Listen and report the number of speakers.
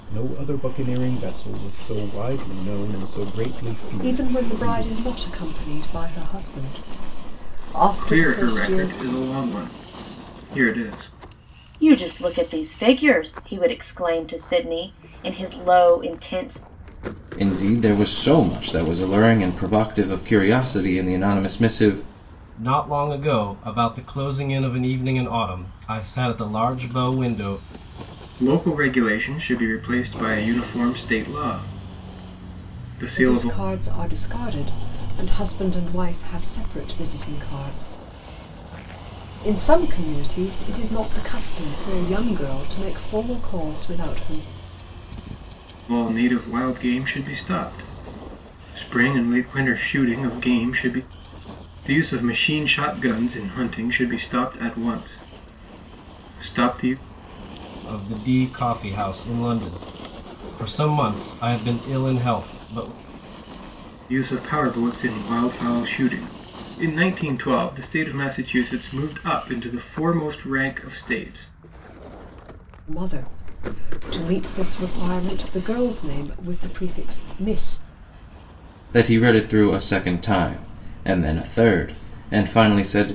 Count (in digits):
6